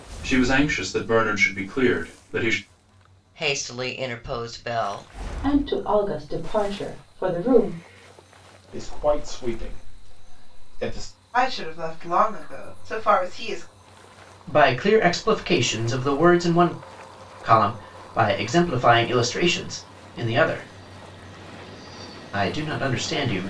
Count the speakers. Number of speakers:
six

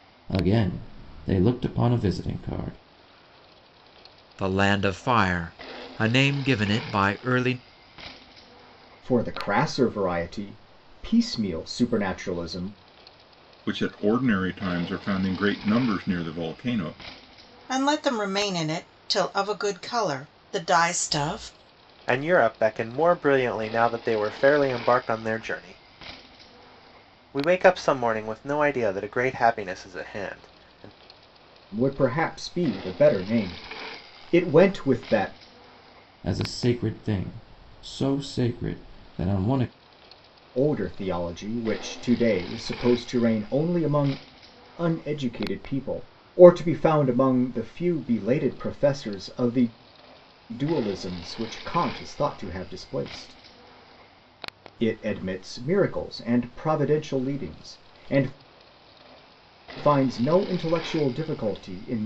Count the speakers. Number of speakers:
six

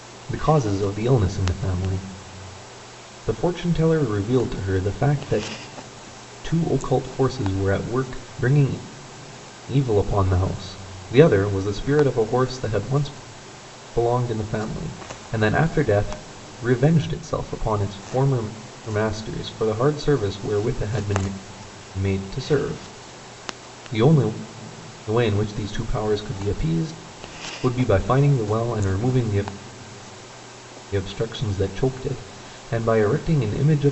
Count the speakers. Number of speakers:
one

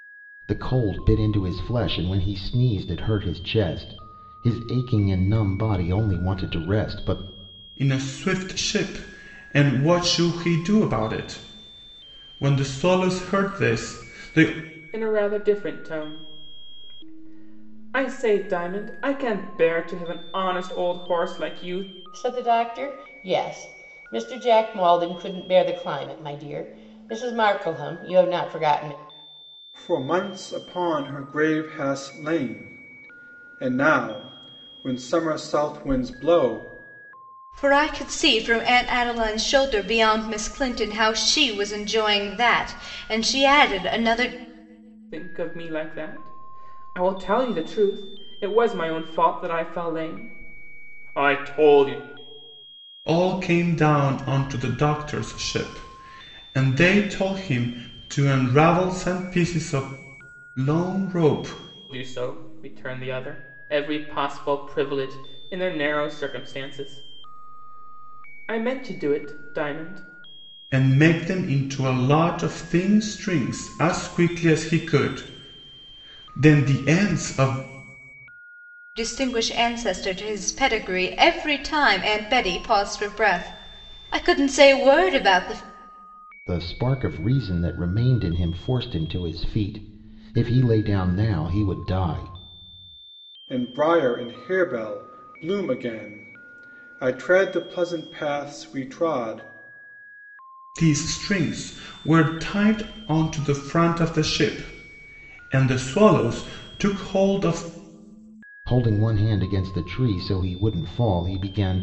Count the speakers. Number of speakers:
six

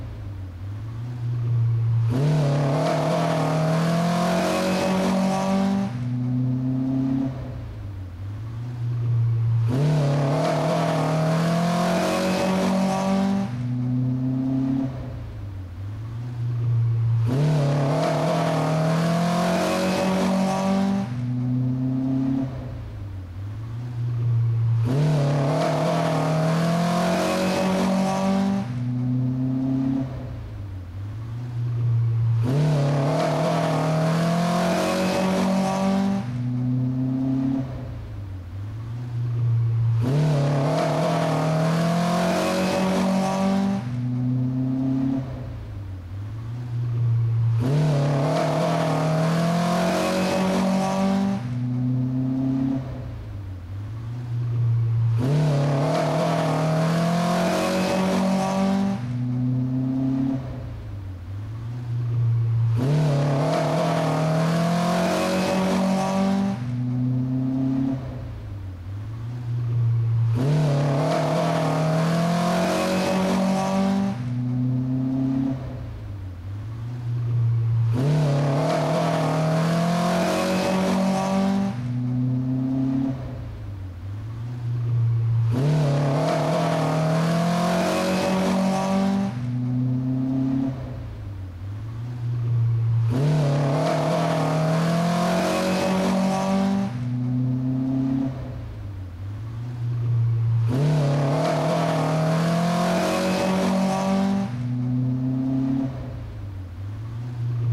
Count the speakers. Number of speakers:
zero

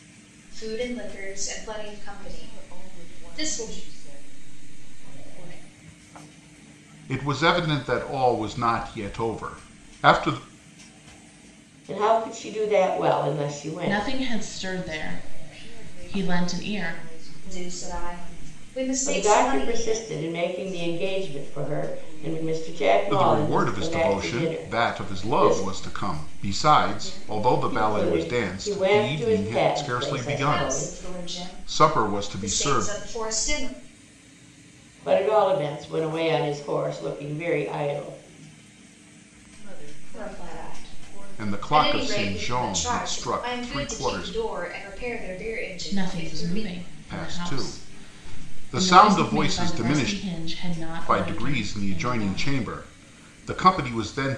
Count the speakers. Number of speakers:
five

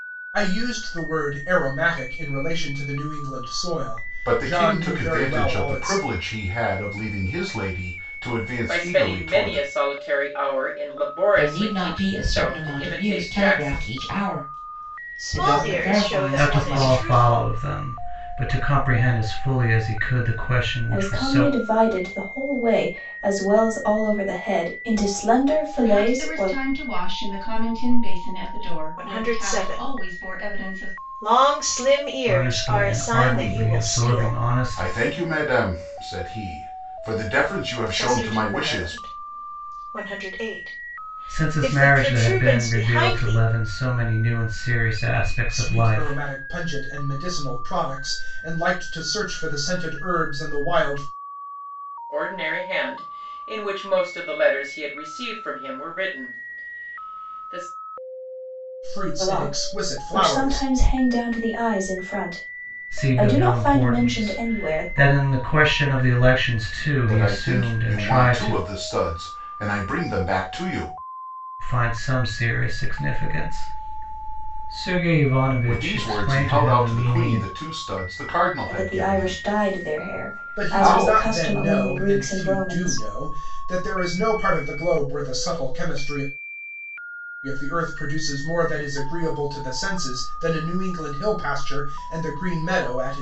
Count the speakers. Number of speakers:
eight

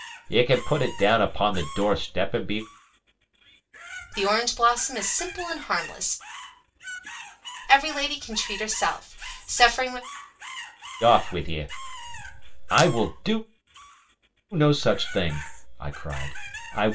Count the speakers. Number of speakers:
two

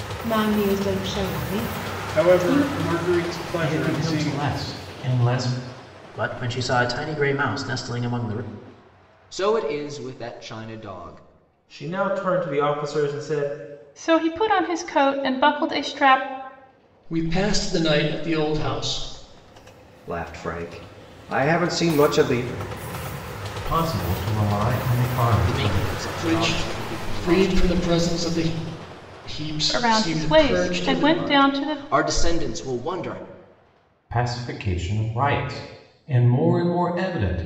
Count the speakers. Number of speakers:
nine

